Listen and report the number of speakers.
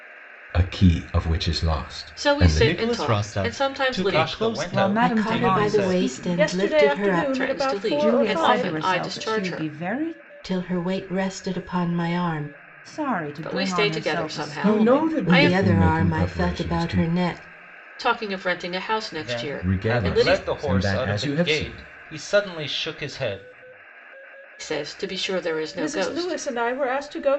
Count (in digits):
7